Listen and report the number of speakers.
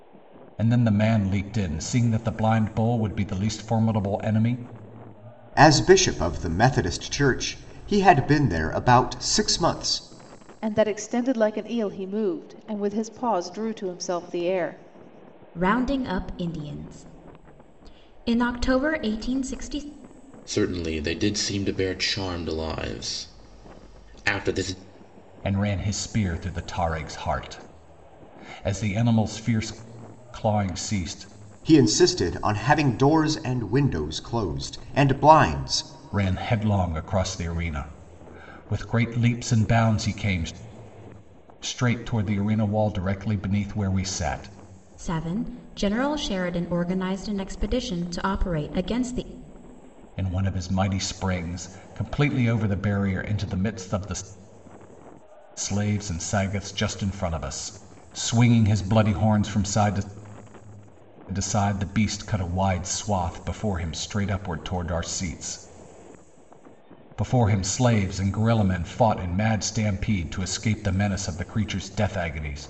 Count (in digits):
5